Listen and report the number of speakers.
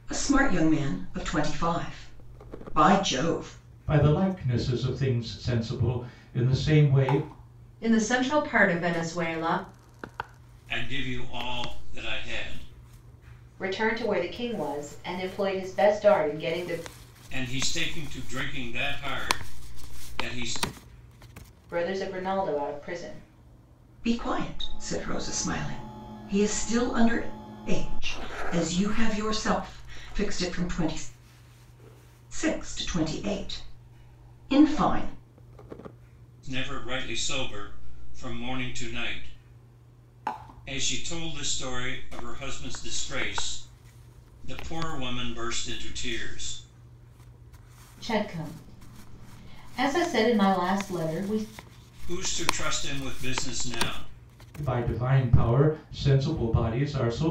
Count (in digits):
5